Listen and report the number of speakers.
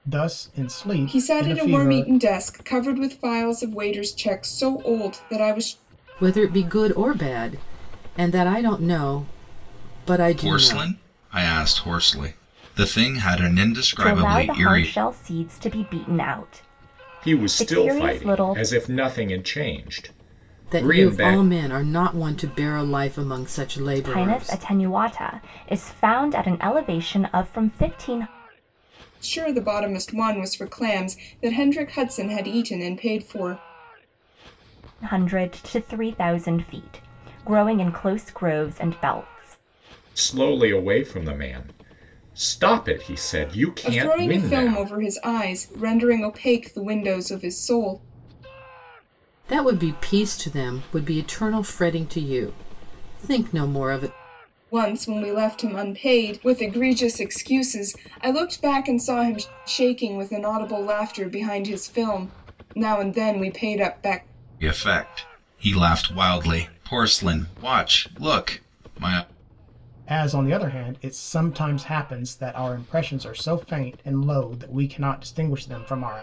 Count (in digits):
6